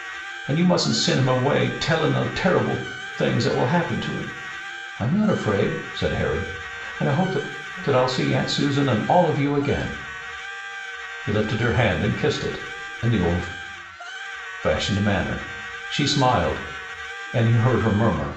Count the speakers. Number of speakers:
1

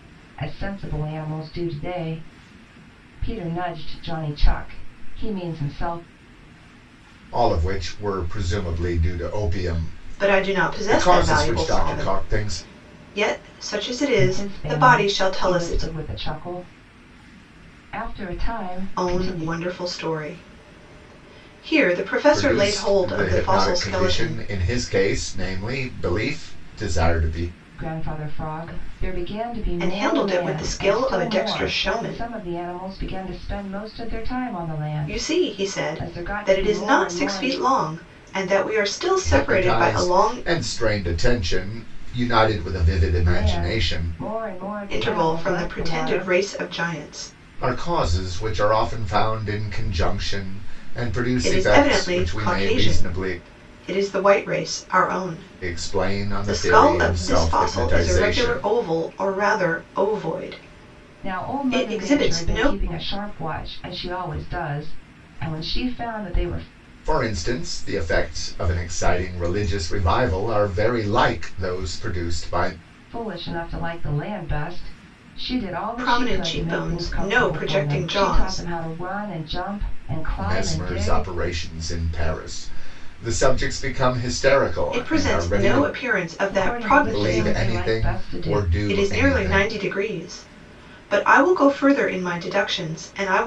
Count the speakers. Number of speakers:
3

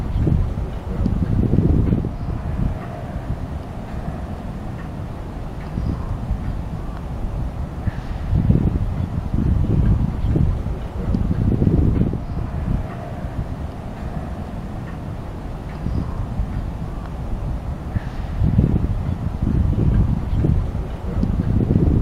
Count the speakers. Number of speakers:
0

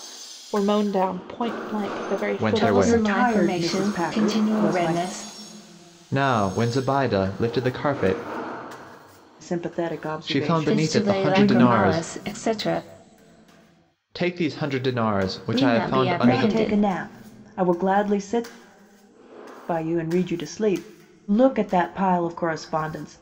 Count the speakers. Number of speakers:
4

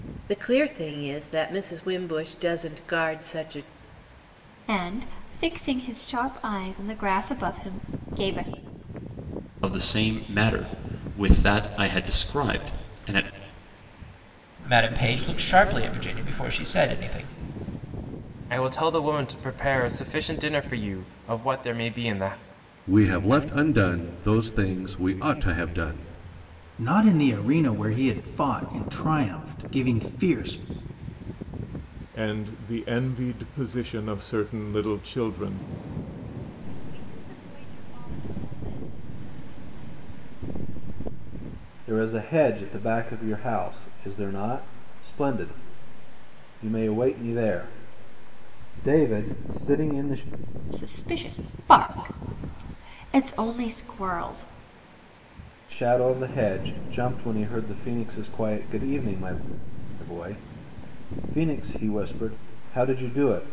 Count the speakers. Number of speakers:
10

